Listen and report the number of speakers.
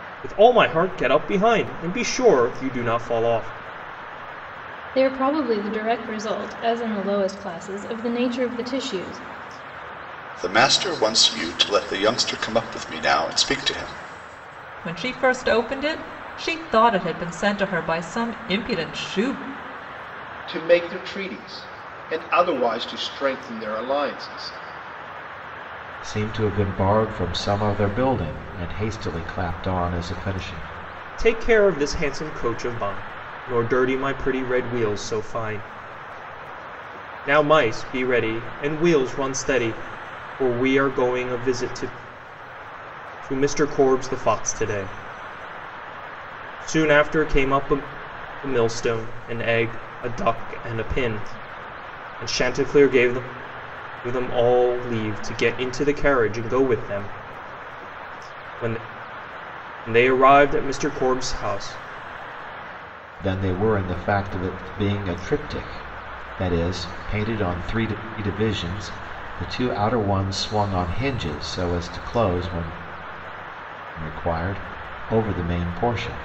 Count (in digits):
6